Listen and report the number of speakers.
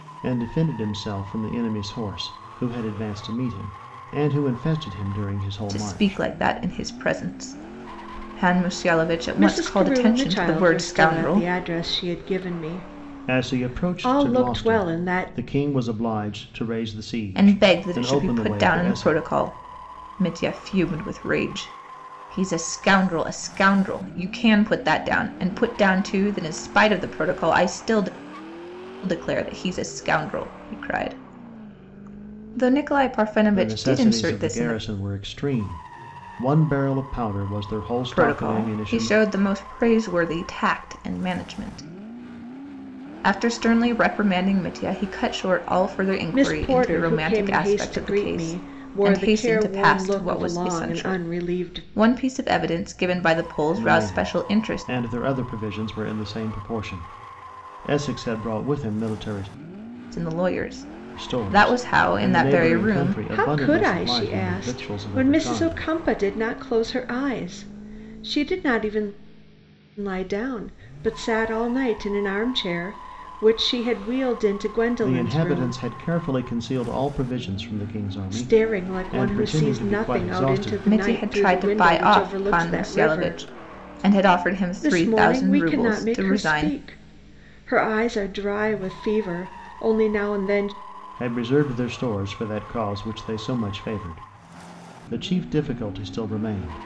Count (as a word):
three